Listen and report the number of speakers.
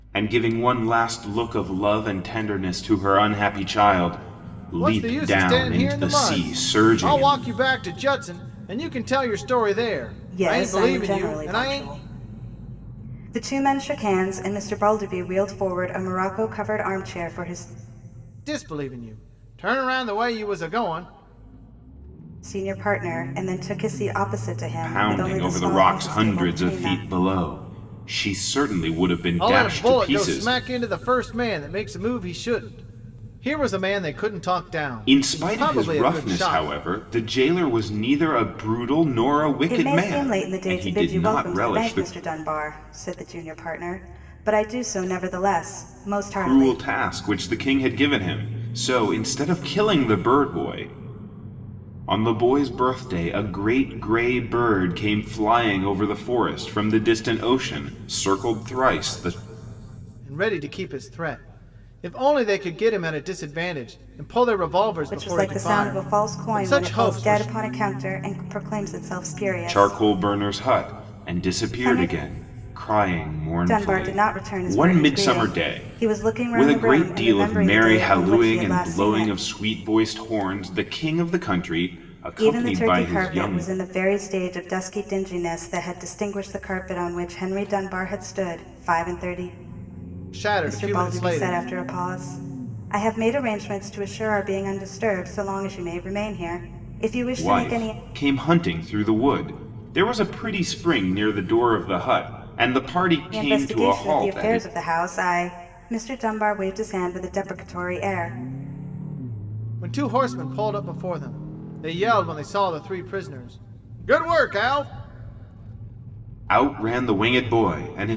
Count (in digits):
3